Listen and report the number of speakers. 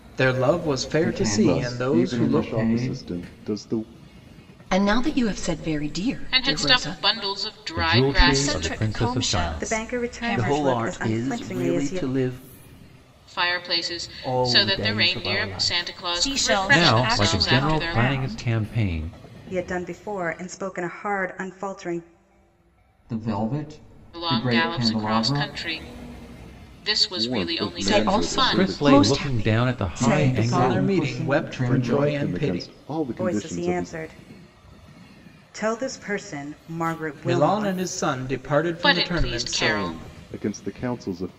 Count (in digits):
9